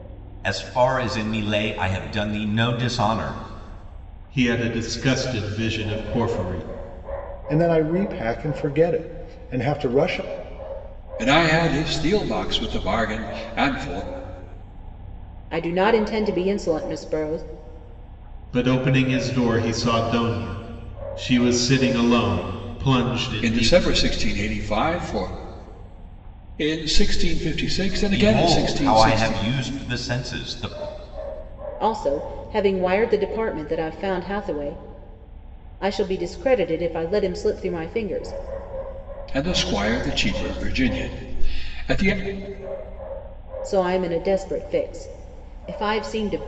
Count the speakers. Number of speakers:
5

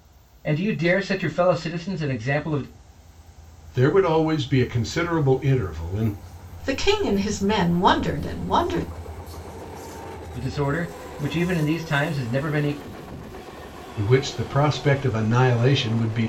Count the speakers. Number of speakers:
3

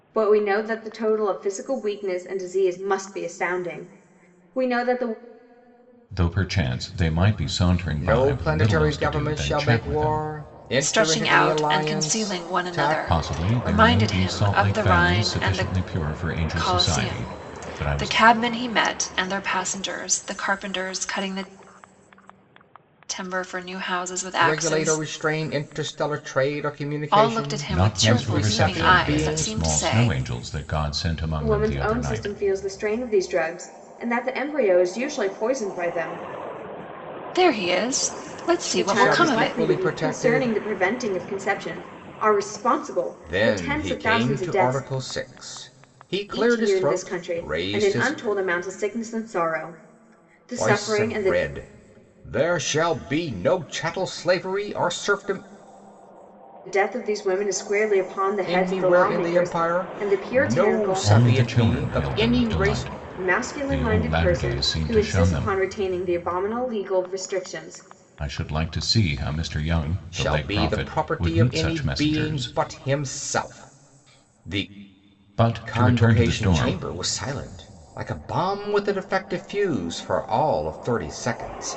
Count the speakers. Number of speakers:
4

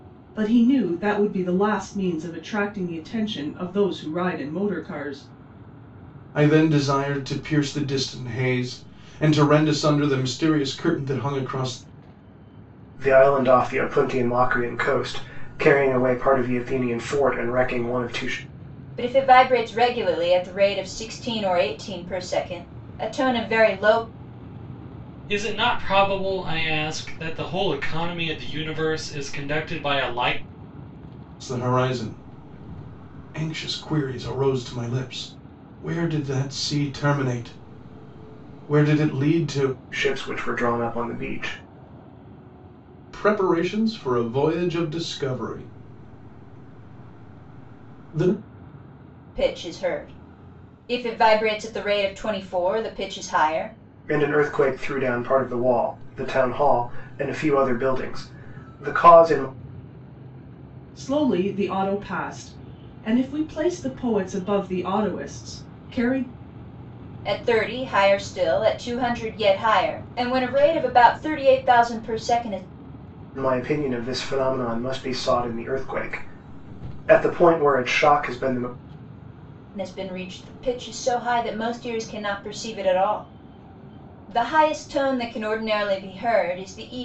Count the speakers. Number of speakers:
5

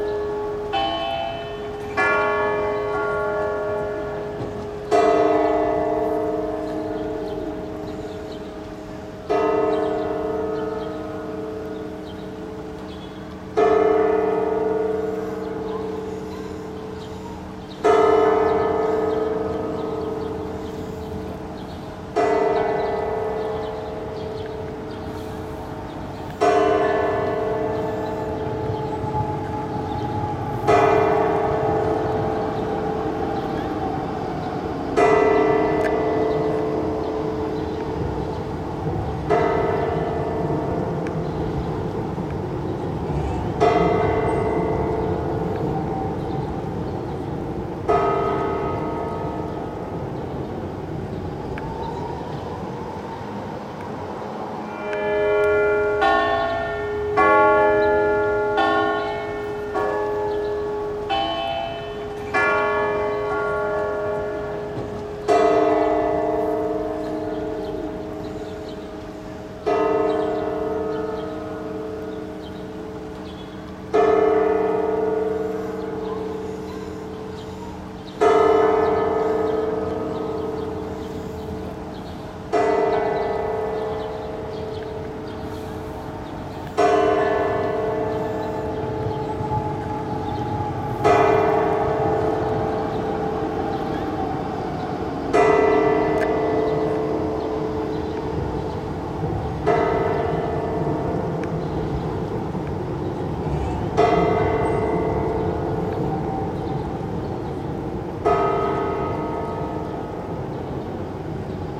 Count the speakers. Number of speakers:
0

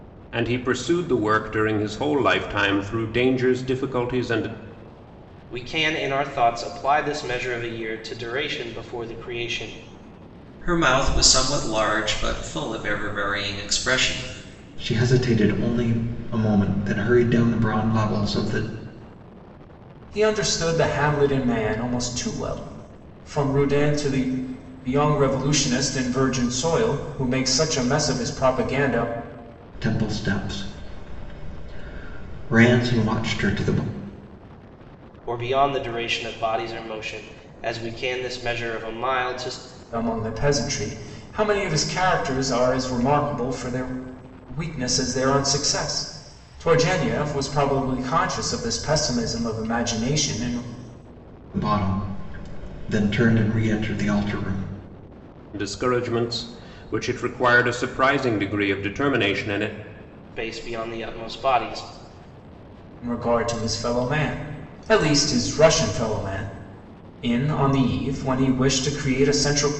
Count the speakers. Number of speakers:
5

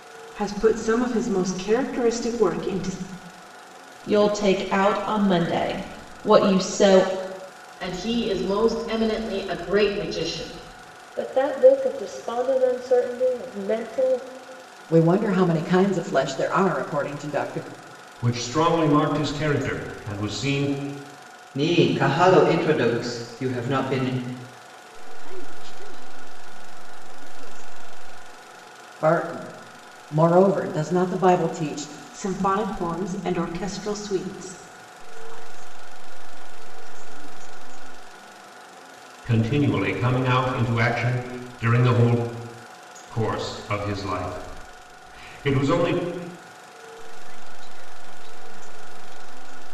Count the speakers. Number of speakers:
8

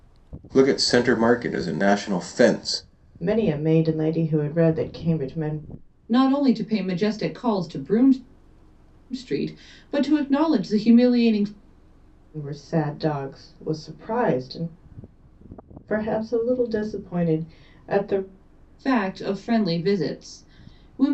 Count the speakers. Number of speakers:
3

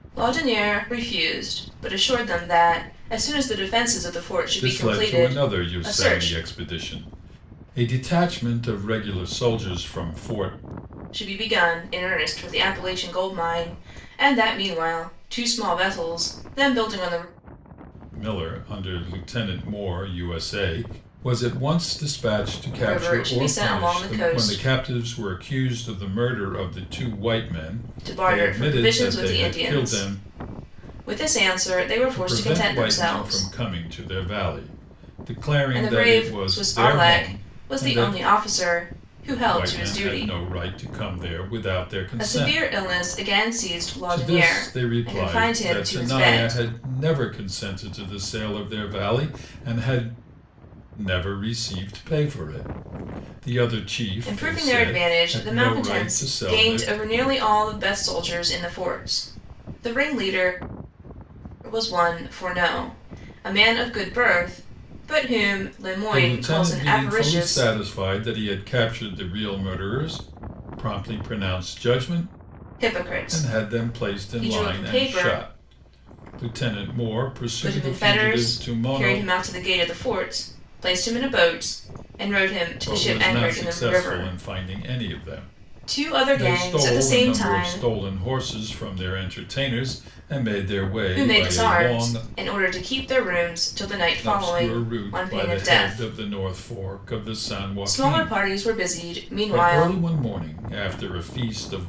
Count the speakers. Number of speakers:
2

